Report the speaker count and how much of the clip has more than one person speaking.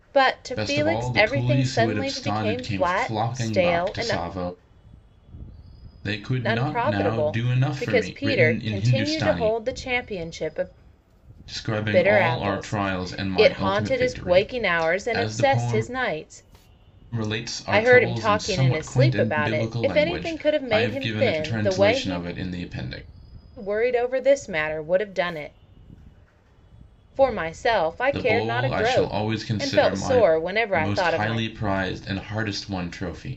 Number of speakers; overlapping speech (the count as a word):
two, about 54%